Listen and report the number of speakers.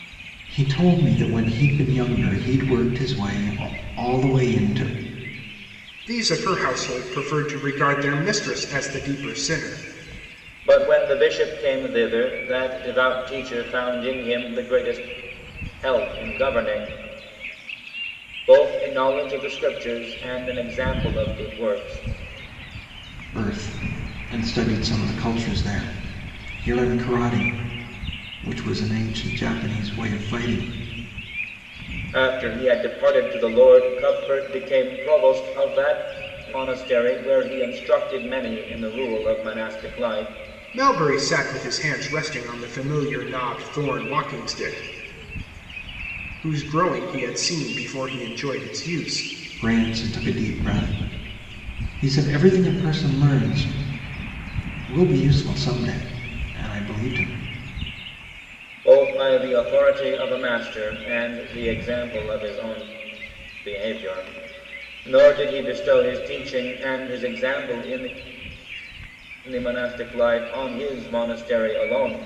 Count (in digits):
3